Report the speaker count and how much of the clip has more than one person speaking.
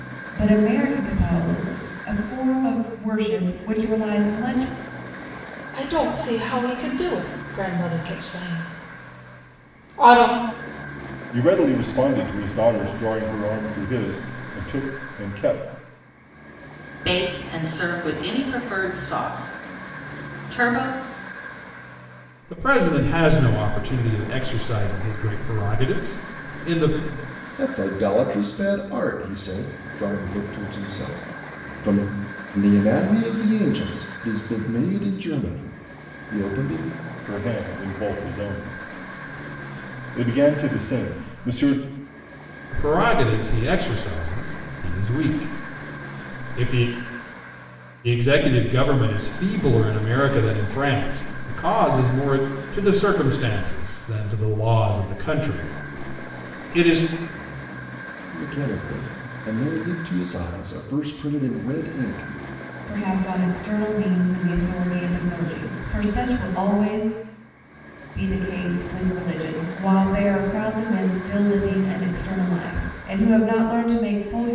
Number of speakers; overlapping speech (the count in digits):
6, no overlap